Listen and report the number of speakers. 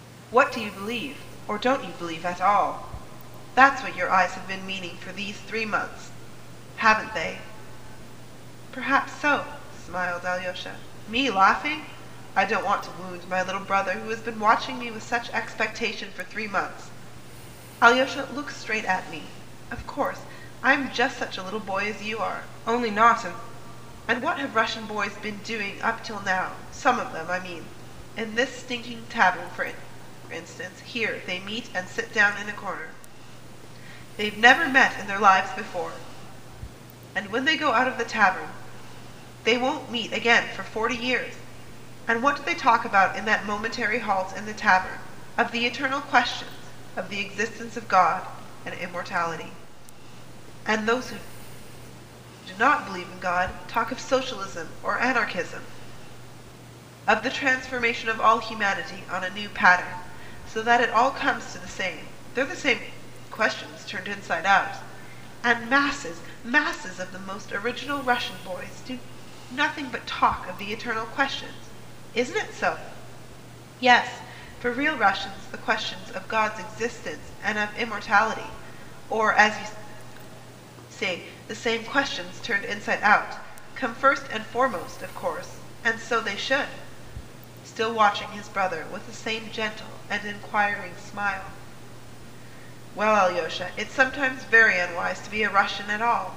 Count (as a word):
one